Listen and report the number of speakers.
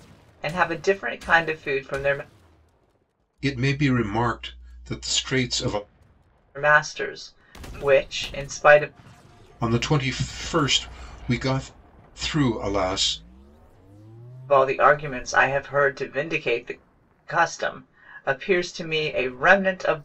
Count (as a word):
two